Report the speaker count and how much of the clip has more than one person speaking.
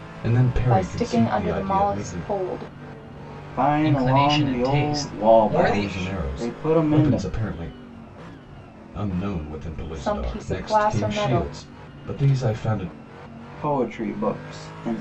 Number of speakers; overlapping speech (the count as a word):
four, about 45%